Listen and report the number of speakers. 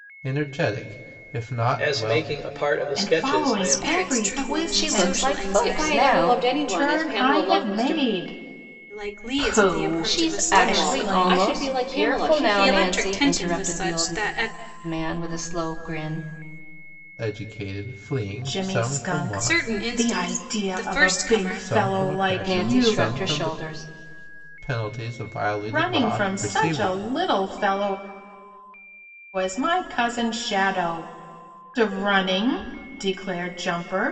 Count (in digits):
6